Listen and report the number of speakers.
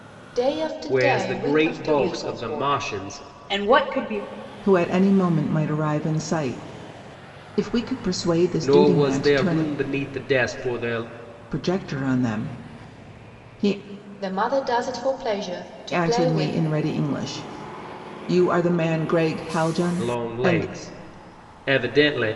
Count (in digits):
4